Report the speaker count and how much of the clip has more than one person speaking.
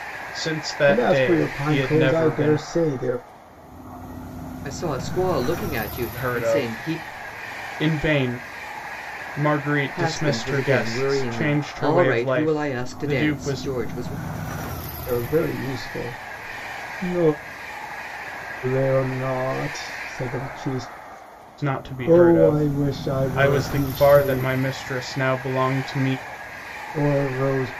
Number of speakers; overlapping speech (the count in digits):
3, about 32%